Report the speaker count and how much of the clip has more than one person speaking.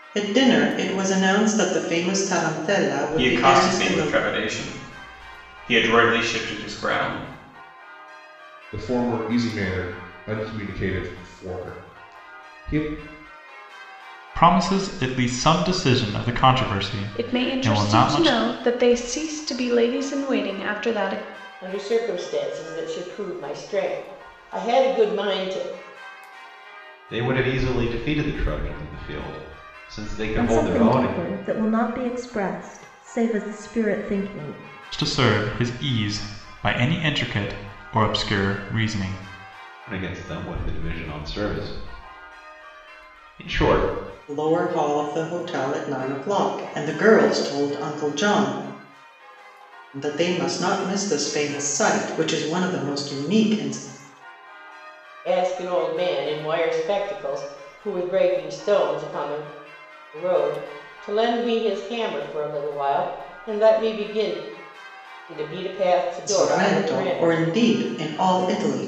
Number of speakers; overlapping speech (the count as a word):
eight, about 6%